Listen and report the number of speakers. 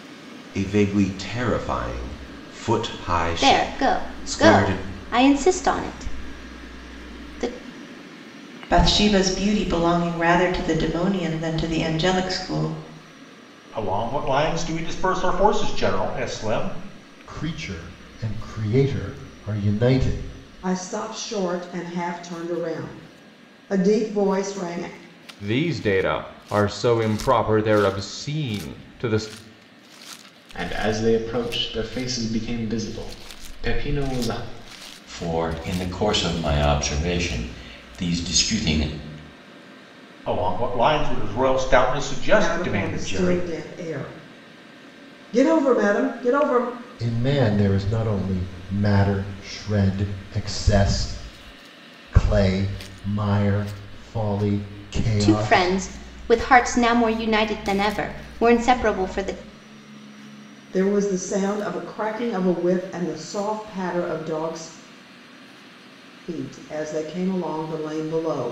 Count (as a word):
nine